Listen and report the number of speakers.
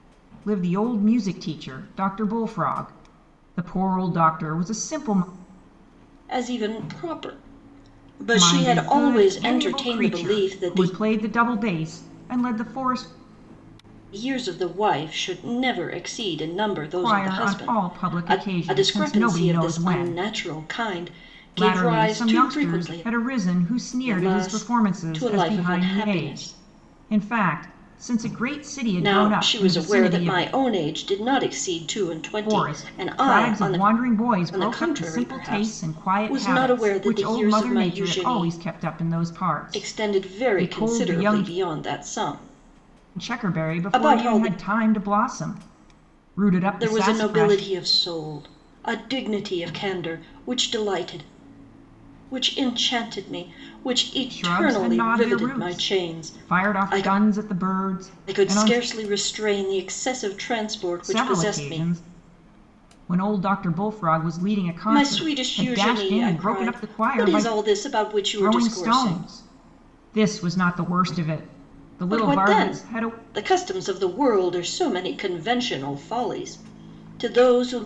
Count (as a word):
two